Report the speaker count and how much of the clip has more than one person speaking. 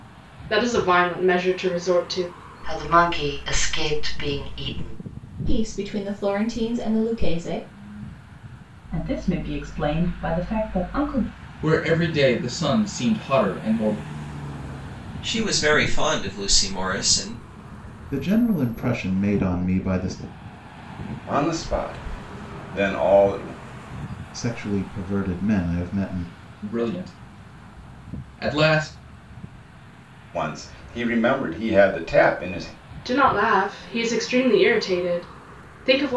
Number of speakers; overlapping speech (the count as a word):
eight, no overlap